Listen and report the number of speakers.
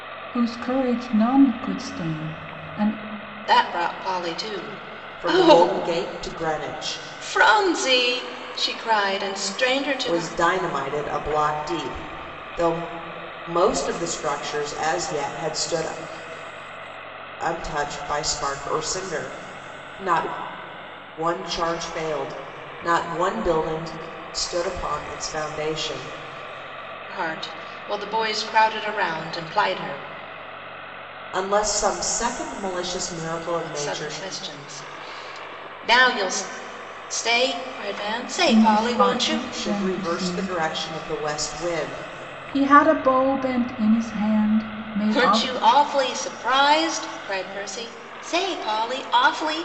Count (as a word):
three